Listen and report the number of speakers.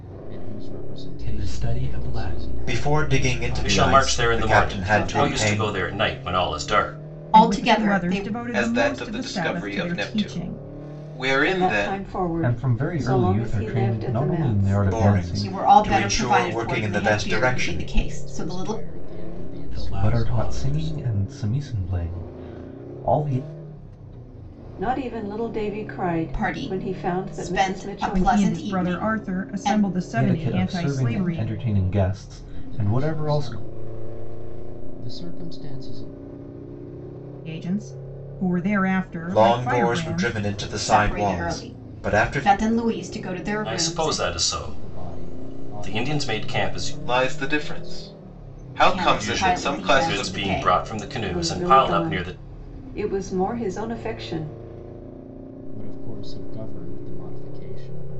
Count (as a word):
nine